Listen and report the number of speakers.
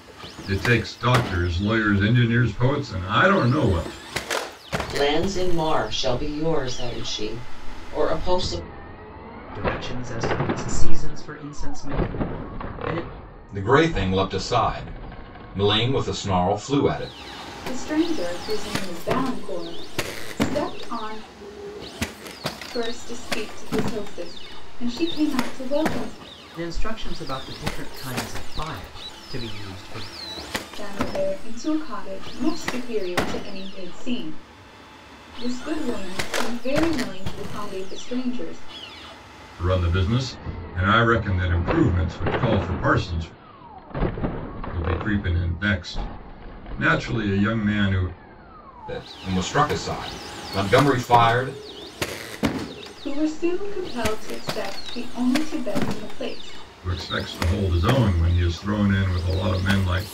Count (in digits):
5